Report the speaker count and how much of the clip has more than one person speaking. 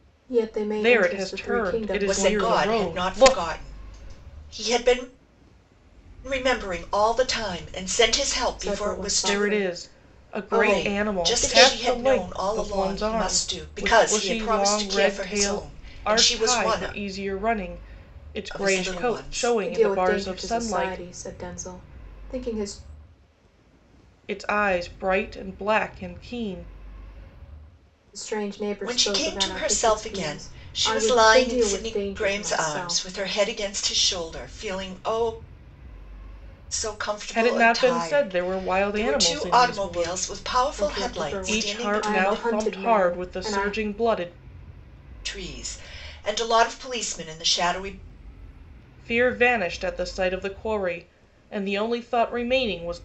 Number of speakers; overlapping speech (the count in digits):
3, about 44%